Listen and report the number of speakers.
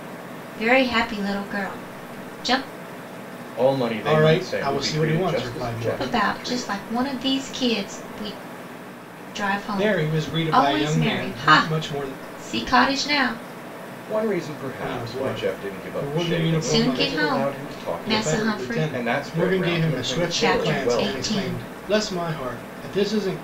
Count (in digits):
3